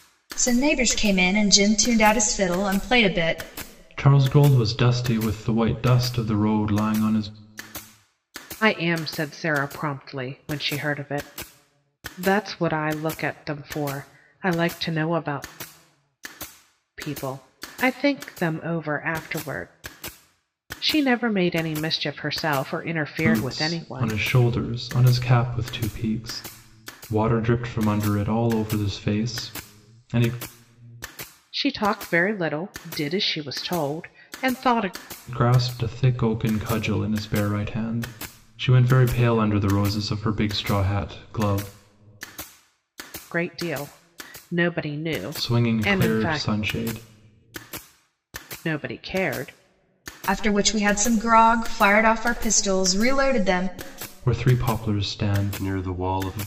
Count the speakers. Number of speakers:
3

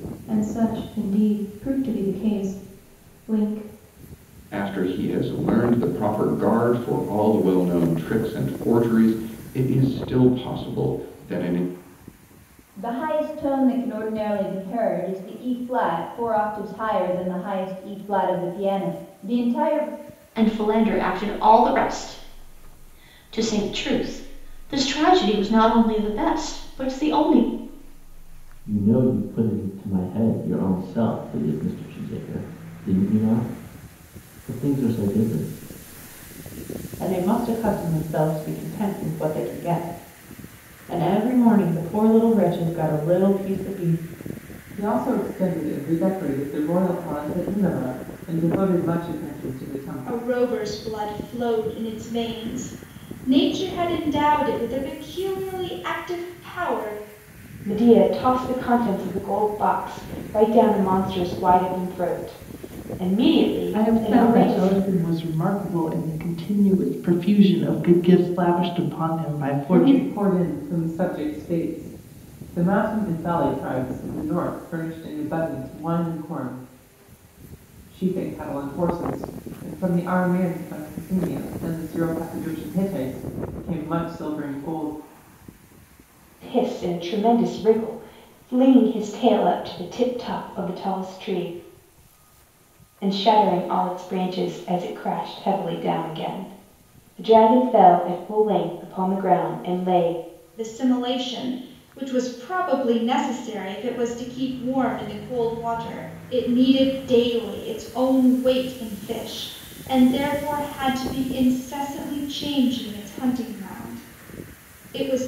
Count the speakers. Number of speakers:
10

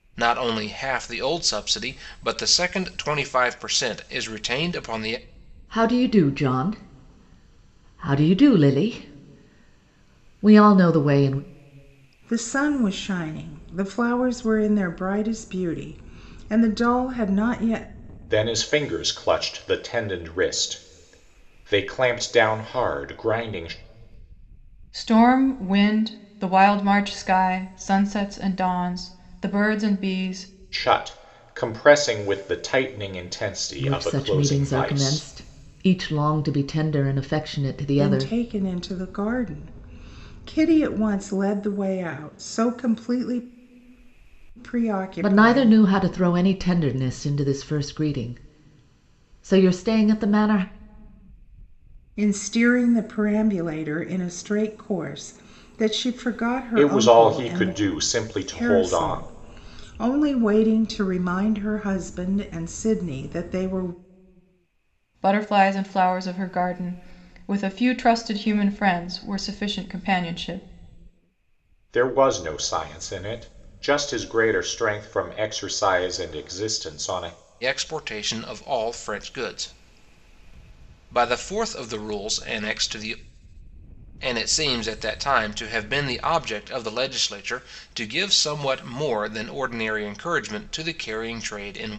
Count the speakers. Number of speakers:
5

